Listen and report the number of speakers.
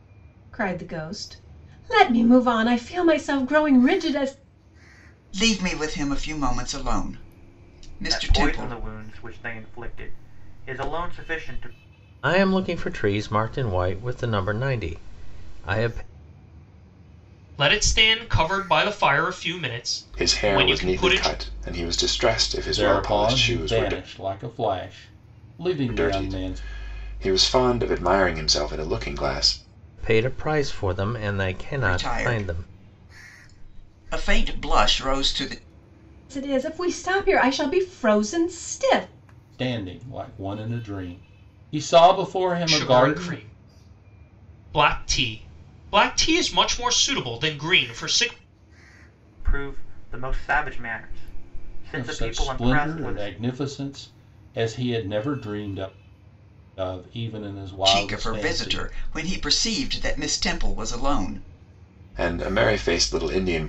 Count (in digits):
7